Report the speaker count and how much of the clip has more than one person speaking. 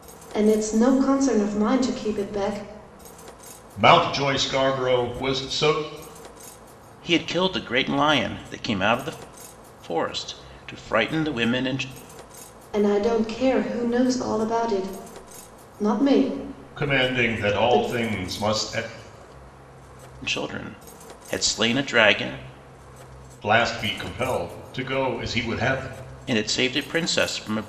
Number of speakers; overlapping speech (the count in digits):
3, about 4%